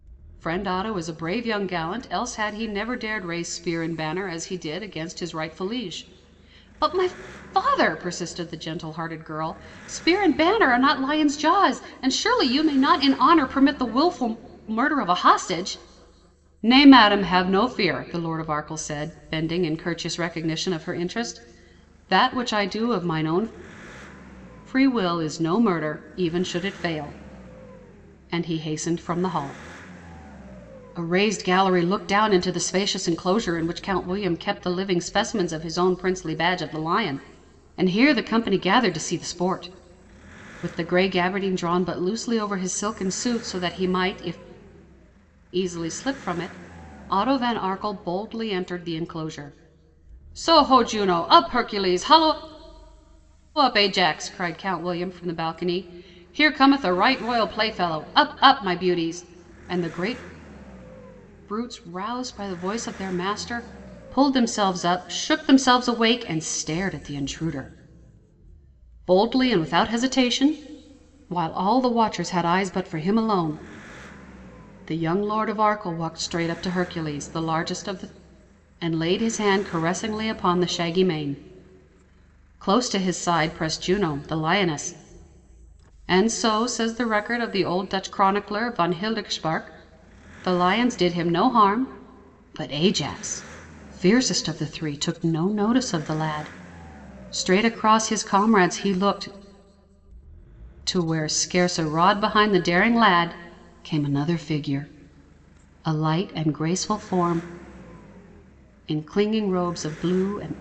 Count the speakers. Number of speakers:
1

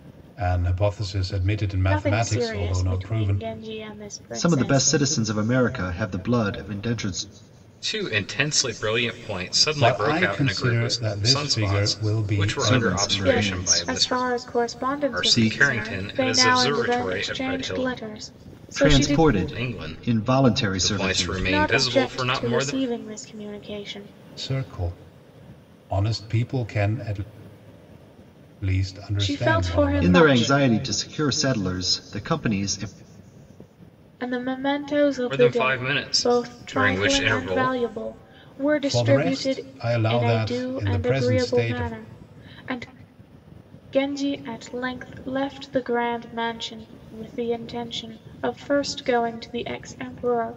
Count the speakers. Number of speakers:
4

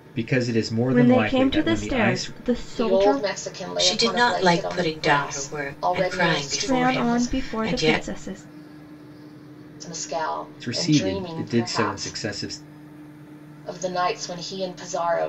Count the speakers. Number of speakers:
4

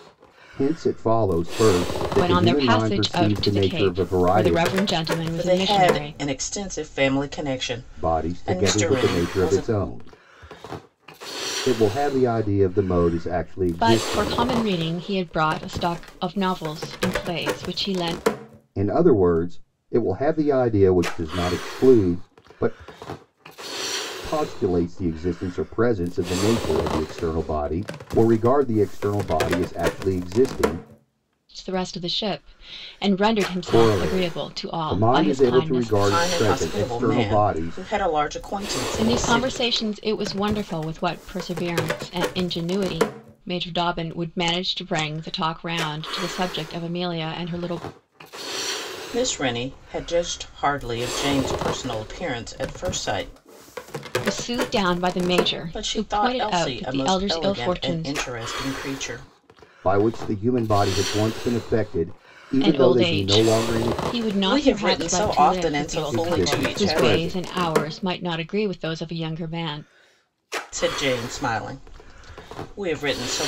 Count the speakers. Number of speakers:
3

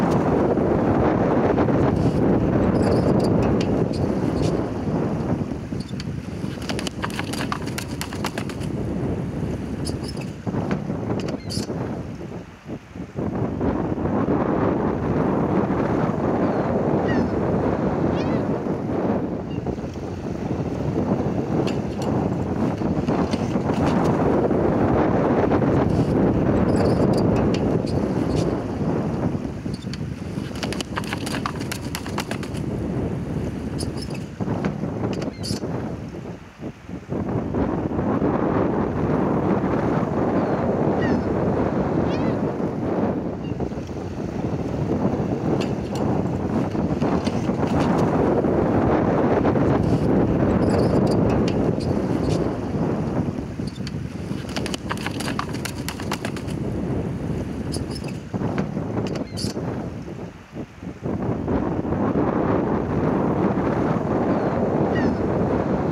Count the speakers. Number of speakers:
0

